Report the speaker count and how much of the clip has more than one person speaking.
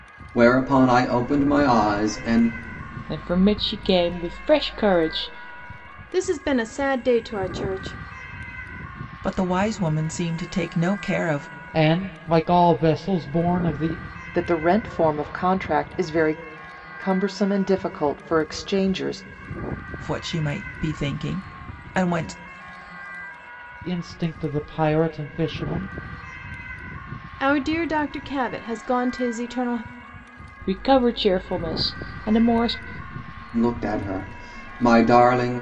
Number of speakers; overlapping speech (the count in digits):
6, no overlap